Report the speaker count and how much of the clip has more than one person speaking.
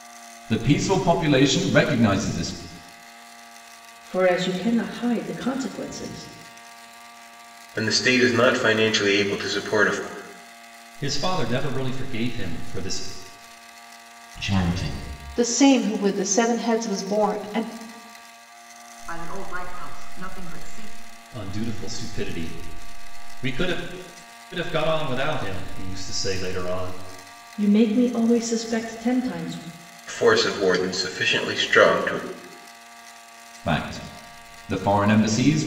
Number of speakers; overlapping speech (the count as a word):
seven, no overlap